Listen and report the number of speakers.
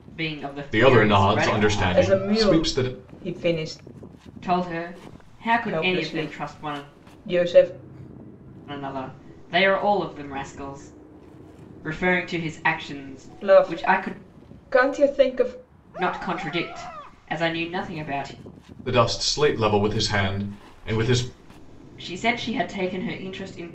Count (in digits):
3